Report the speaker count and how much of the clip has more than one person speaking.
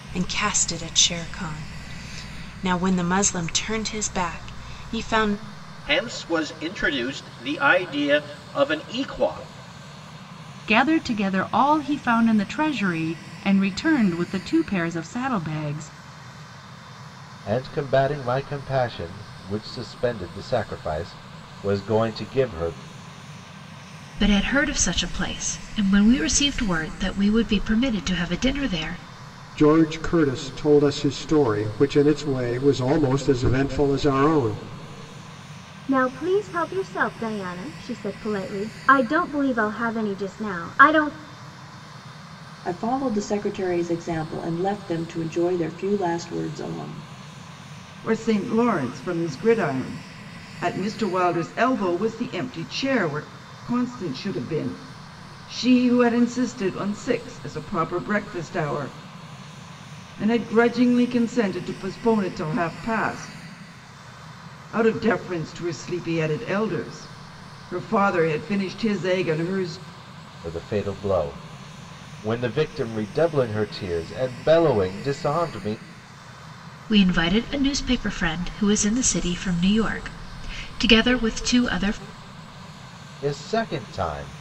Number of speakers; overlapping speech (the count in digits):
9, no overlap